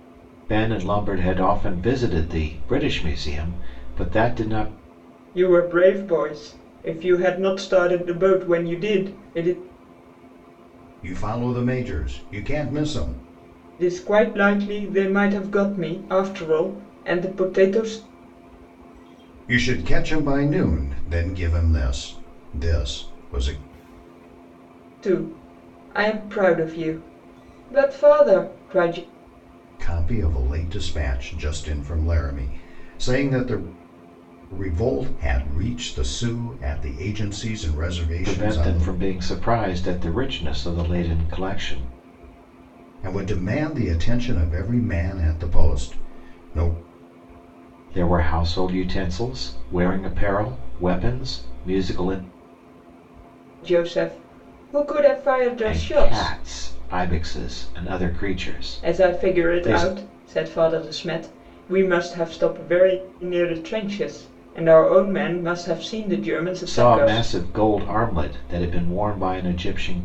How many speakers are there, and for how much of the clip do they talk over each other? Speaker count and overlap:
three, about 4%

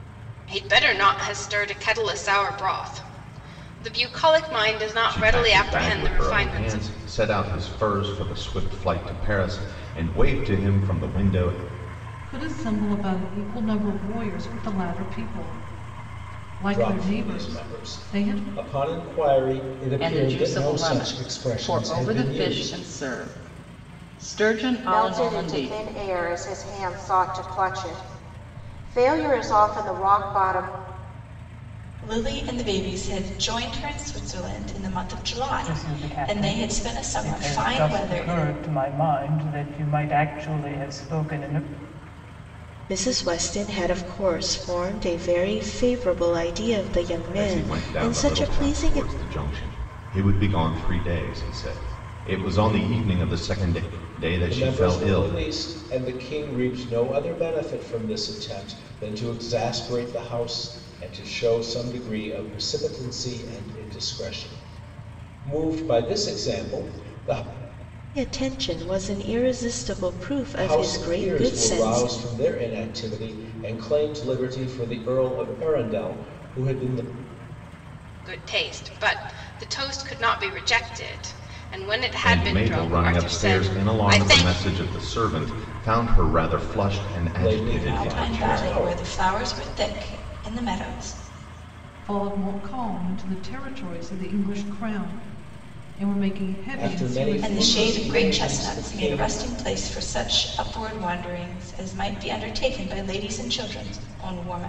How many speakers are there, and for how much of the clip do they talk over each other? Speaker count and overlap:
nine, about 20%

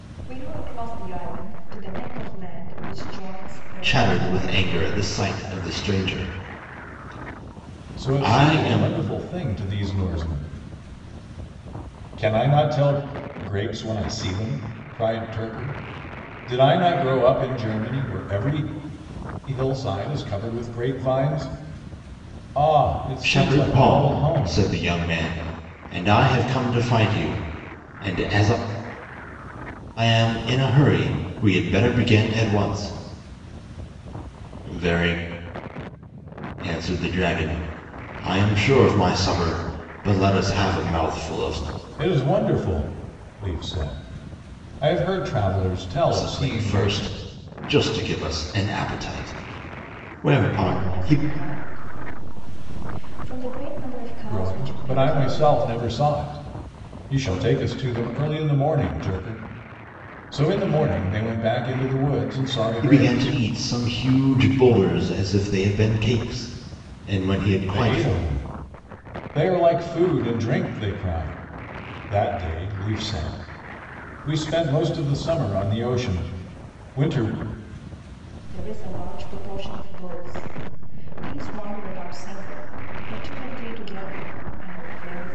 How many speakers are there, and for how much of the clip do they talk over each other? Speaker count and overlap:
three, about 9%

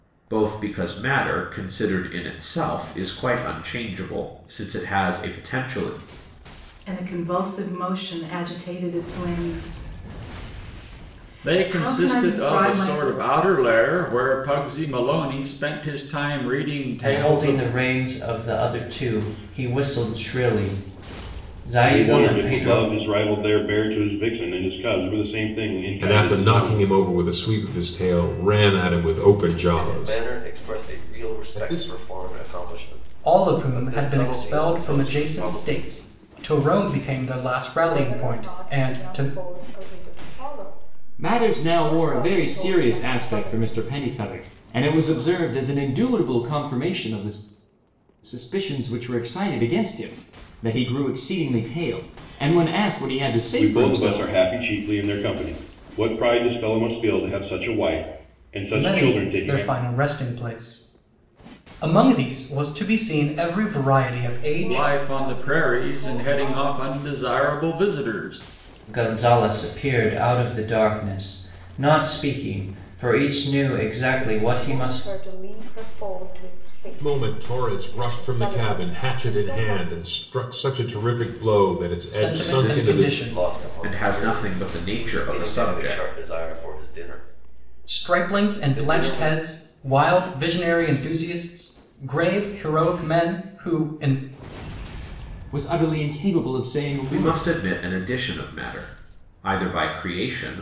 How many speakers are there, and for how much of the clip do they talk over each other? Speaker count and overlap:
ten, about 28%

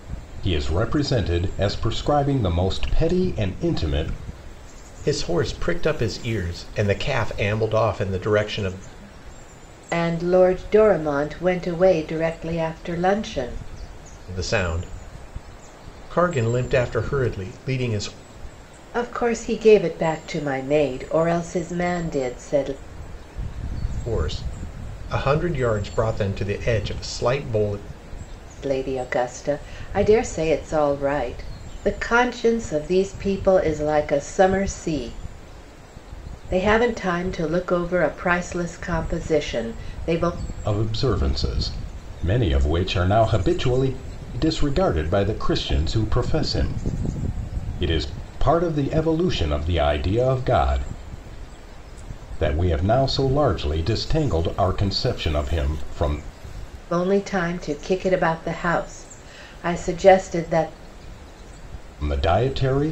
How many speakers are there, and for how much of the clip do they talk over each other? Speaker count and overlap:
three, no overlap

